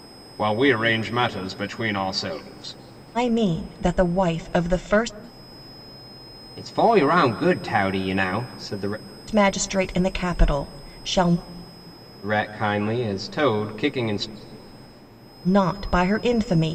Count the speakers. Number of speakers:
two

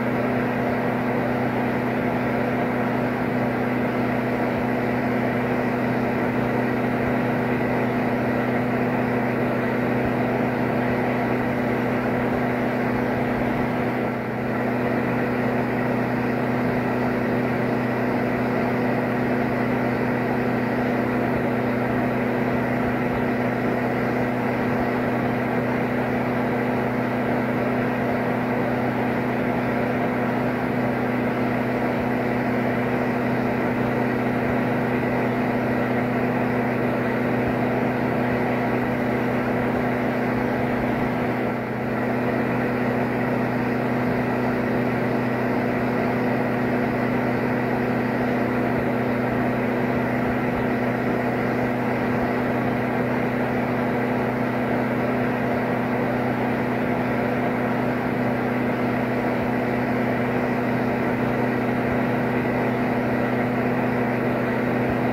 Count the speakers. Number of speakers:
zero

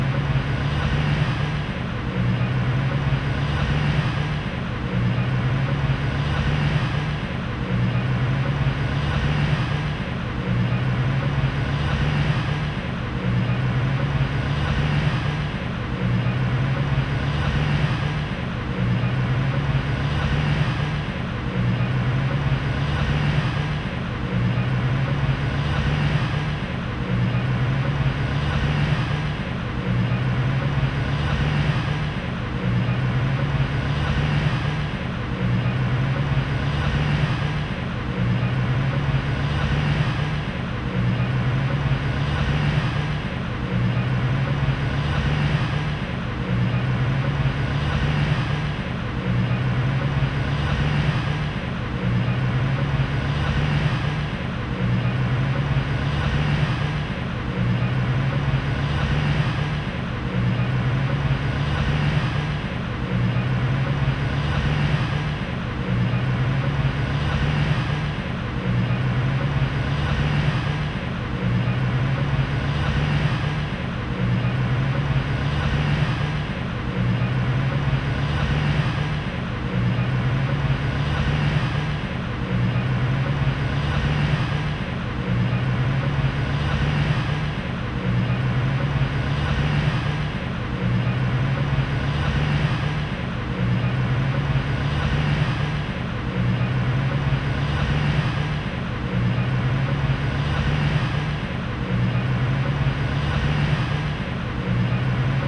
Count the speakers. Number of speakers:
zero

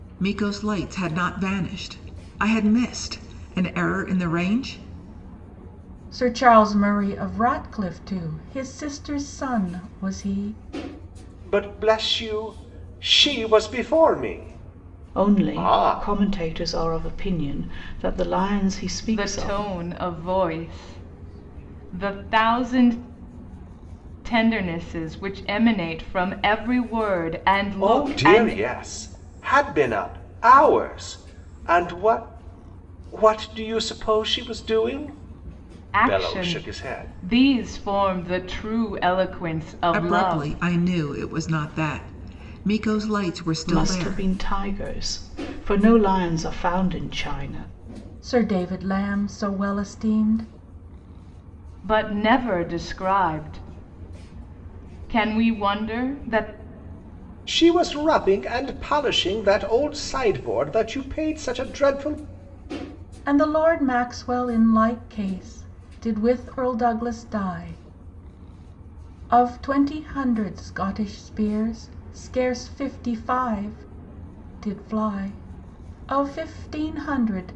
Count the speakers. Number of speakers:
five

